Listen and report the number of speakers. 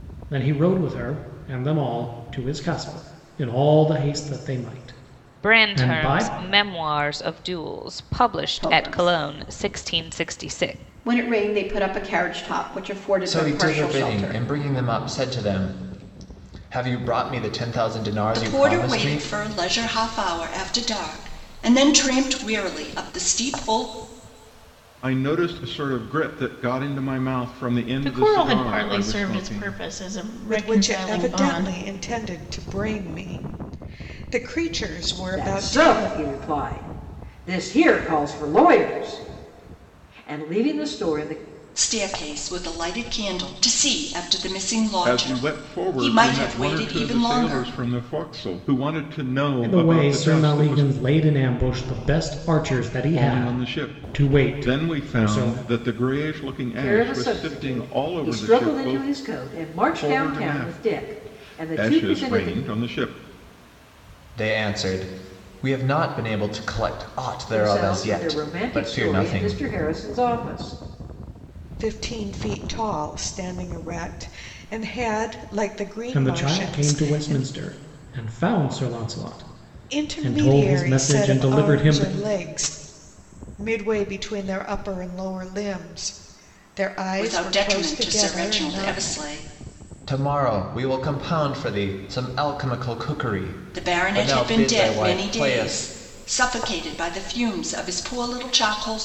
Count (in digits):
9